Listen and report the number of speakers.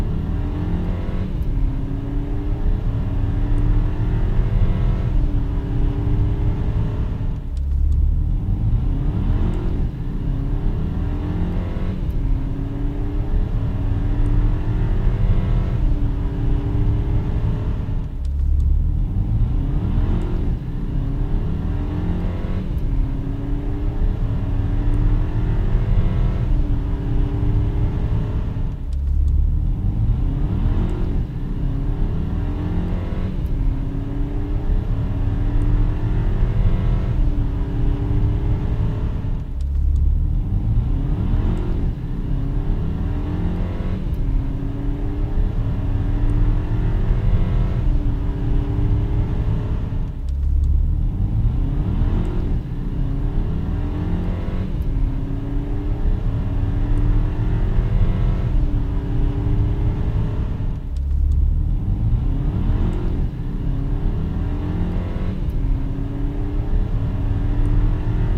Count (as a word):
zero